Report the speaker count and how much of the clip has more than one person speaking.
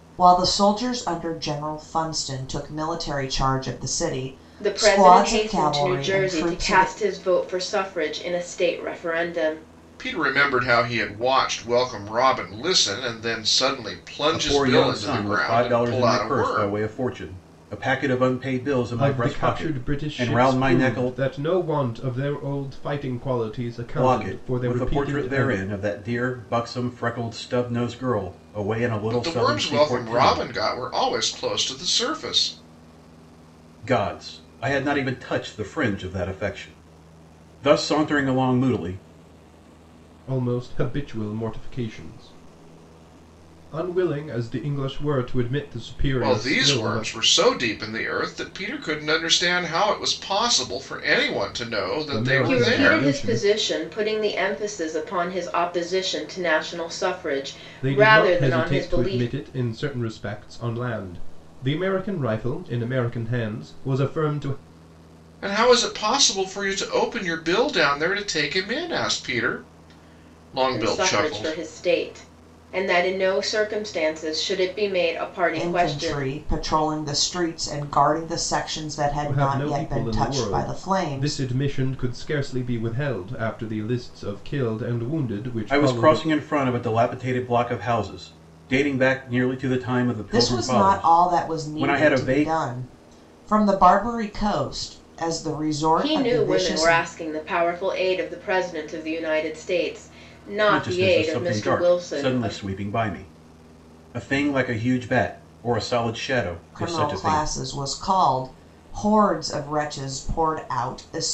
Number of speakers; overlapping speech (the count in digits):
5, about 22%